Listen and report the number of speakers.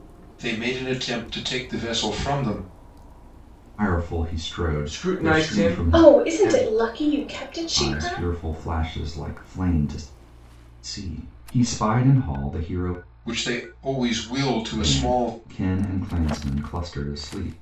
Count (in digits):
4